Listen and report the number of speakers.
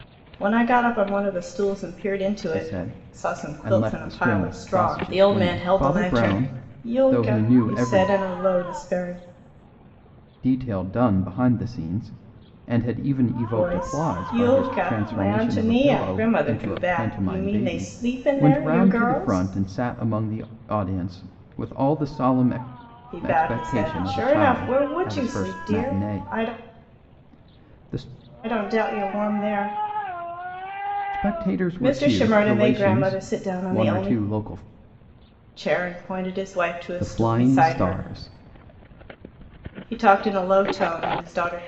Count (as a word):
two